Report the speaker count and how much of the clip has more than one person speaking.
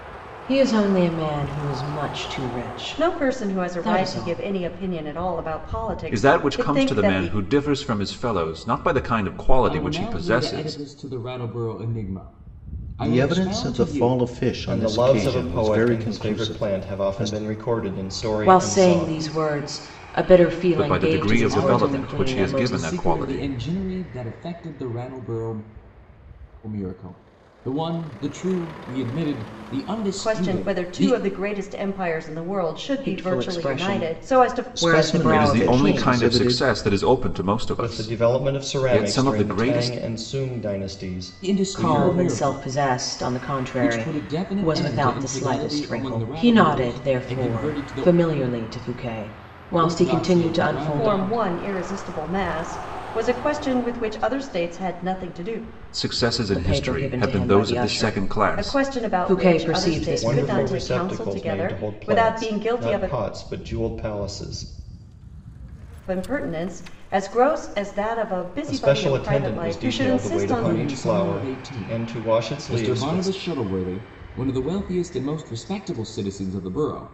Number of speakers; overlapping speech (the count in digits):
6, about 48%